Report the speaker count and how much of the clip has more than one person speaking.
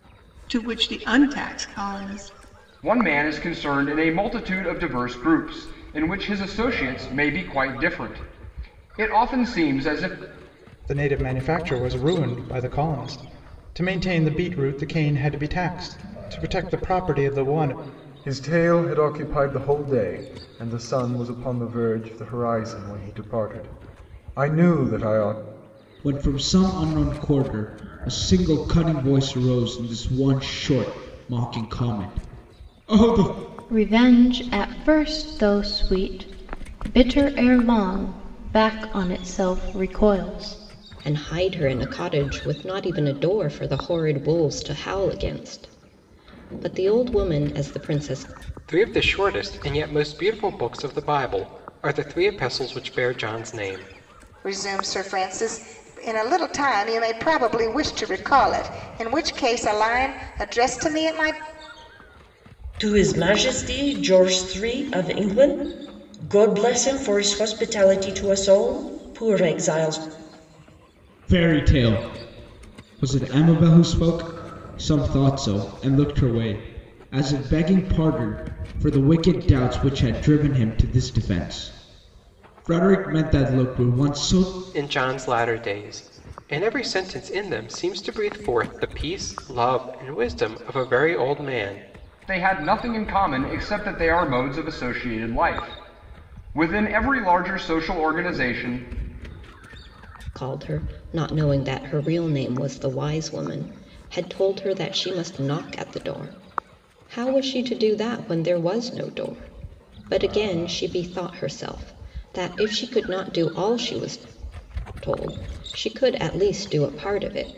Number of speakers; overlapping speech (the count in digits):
10, no overlap